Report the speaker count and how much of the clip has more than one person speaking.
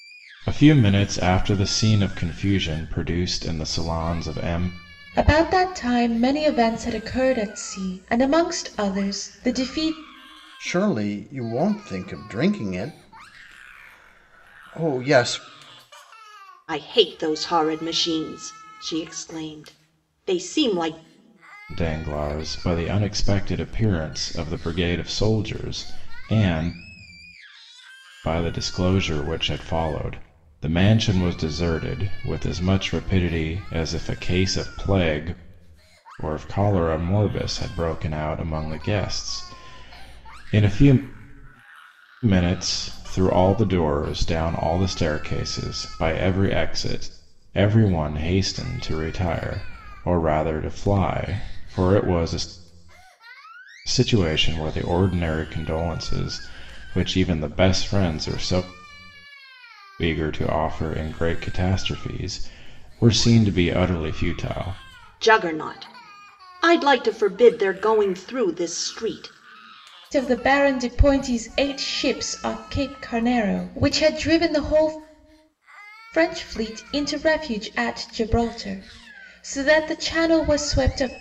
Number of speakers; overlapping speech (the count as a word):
four, no overlap